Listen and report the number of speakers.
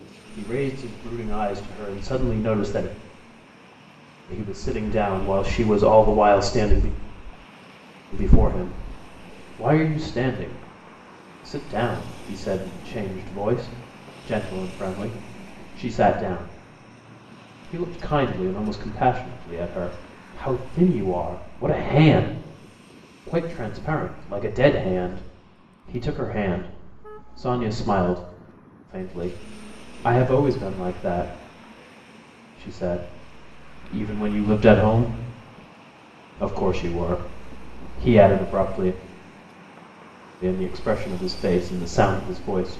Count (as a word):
one